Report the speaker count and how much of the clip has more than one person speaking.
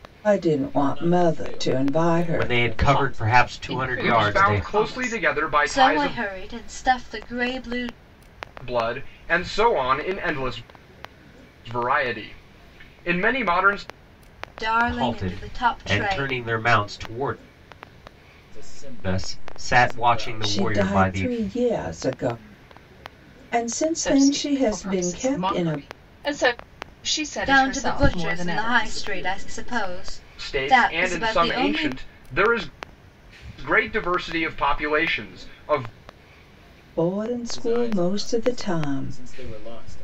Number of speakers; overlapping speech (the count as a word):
six, about 42%